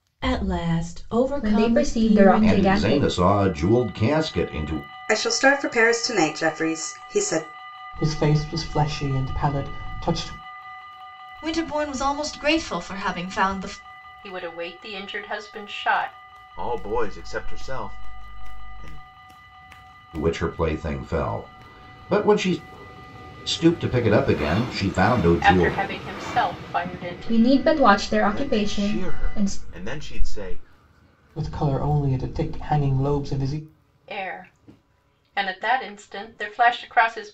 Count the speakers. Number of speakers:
eight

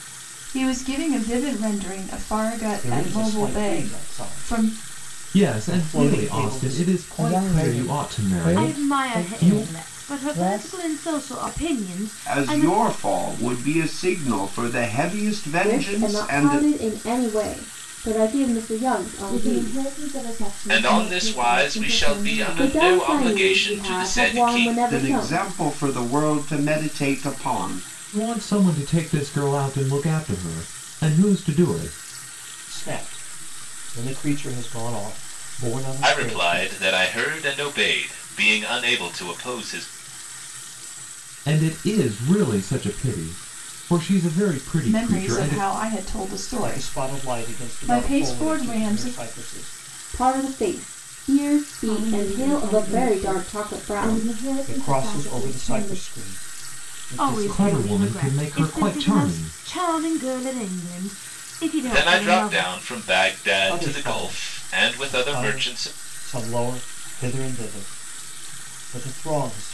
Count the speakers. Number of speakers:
nine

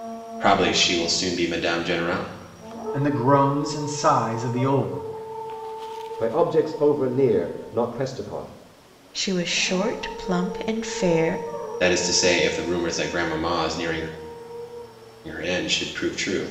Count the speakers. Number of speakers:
four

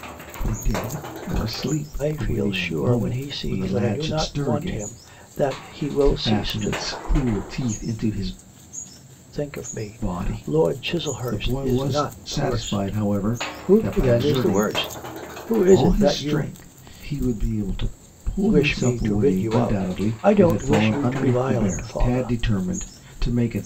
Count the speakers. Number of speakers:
two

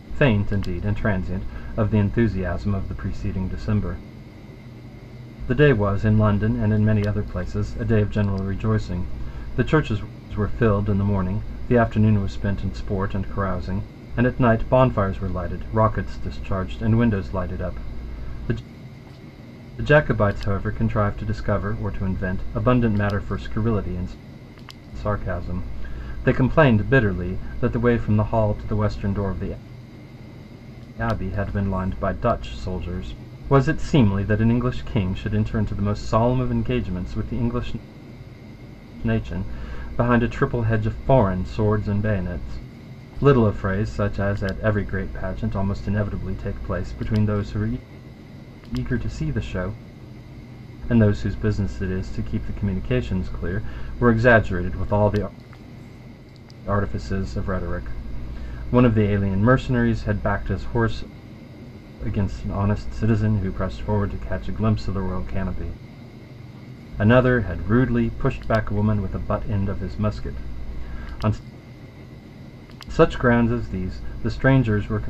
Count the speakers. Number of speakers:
one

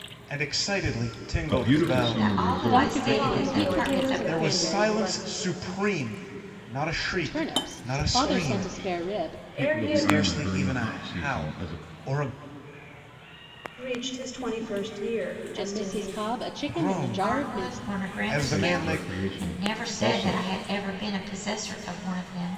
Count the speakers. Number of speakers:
five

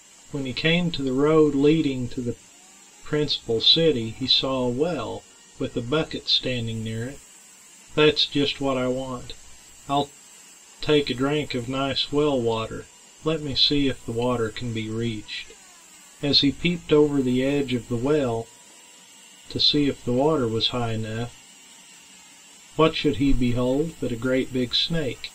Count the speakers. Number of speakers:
one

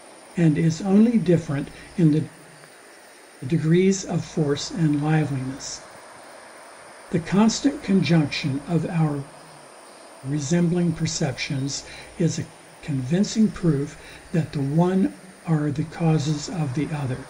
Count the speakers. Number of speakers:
one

